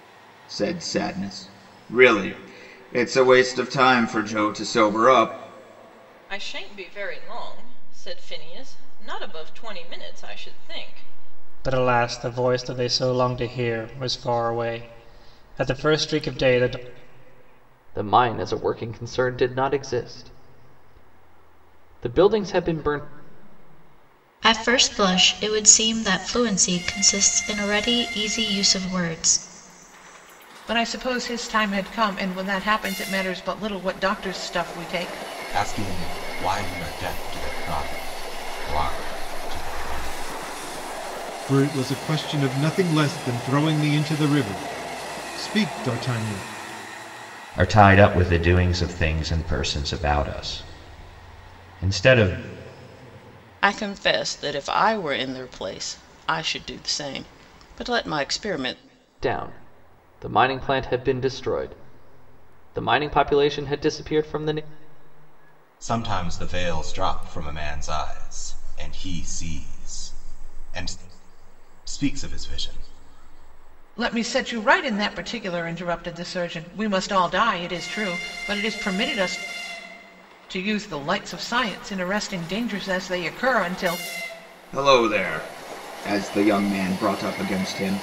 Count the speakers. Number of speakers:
ten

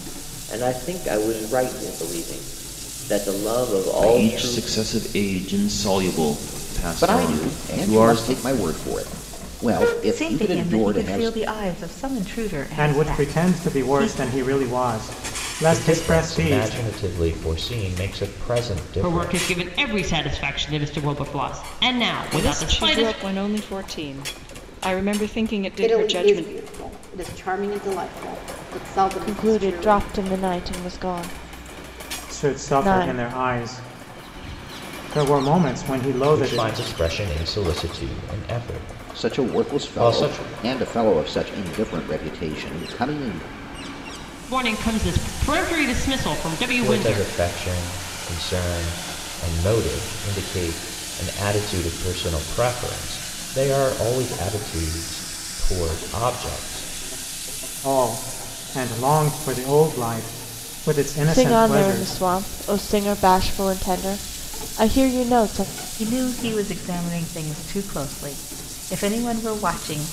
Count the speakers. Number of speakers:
ten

